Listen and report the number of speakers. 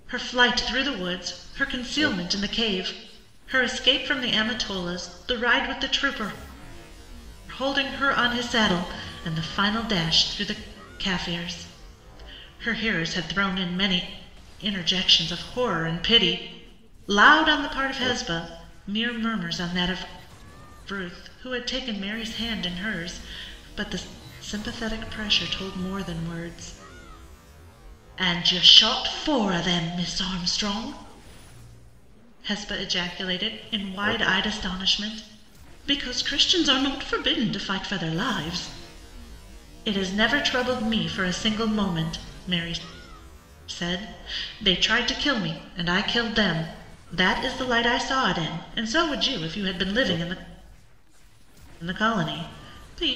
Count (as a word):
one